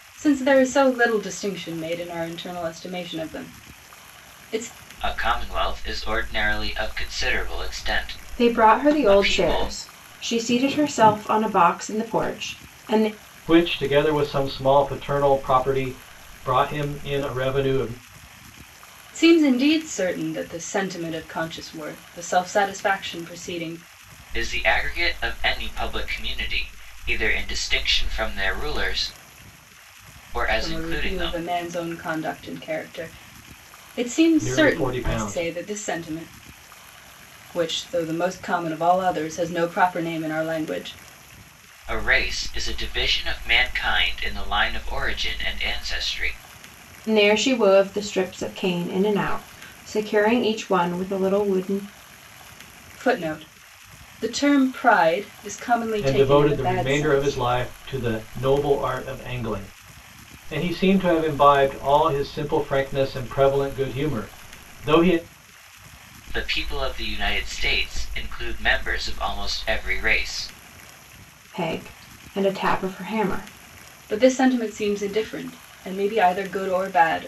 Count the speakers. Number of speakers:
4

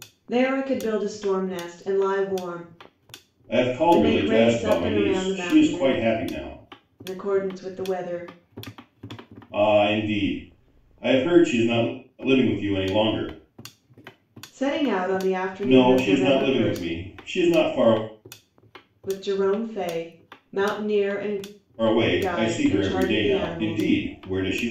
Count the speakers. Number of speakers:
2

